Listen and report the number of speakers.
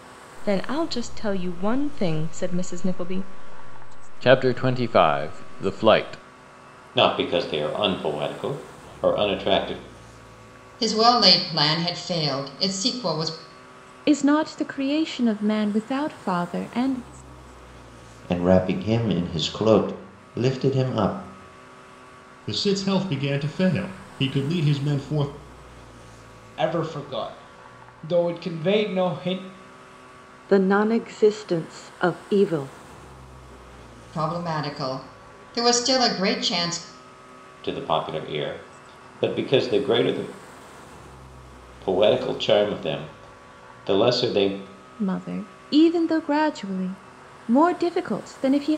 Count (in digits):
9